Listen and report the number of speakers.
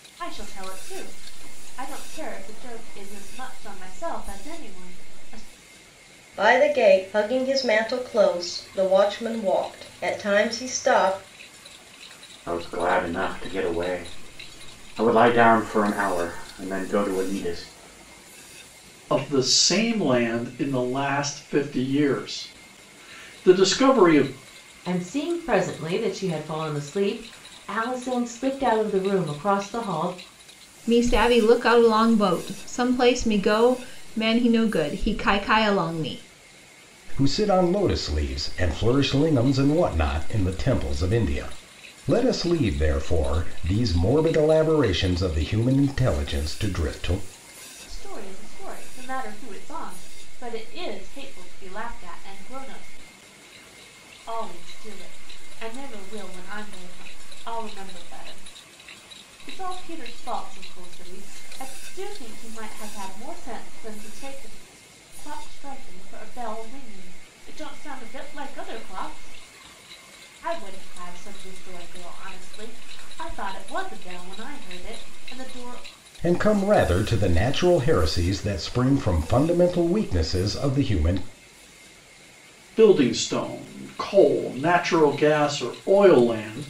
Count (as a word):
seven